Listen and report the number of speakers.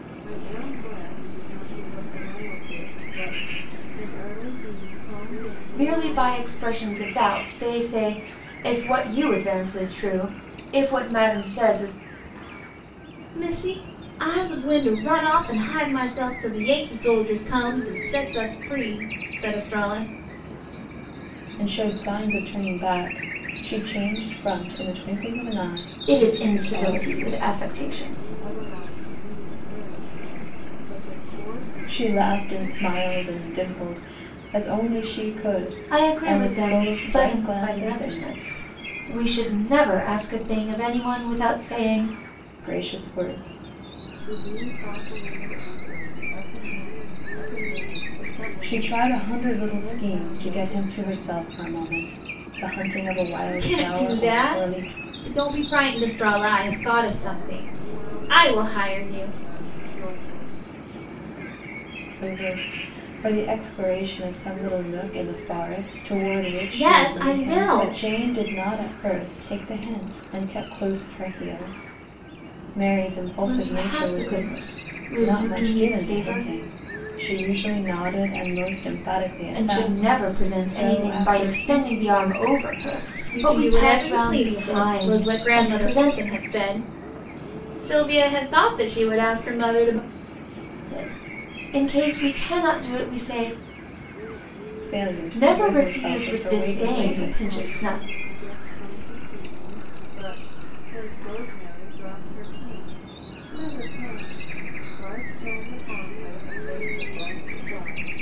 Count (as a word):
four